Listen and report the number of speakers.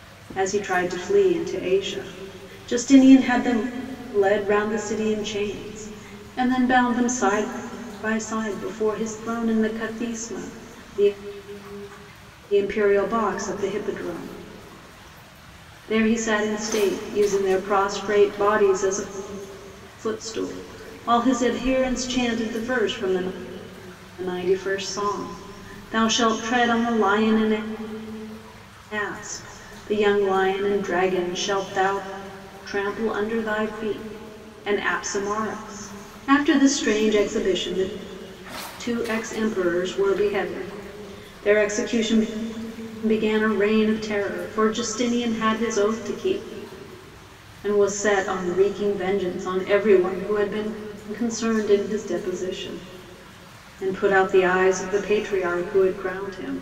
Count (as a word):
one